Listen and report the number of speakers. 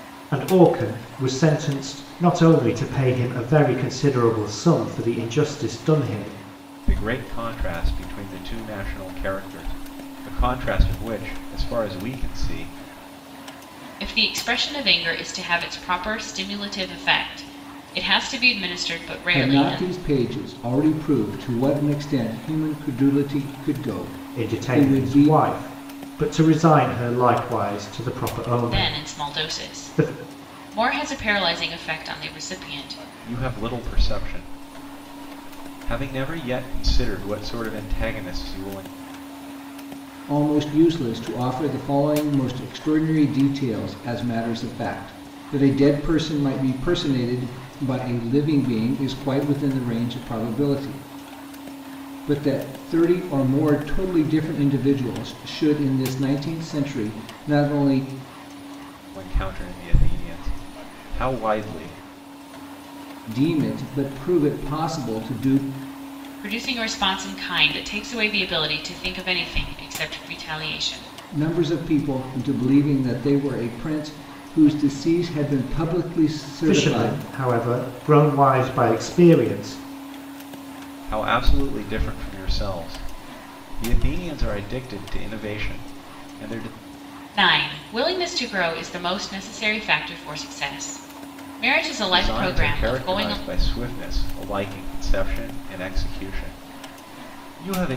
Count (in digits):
4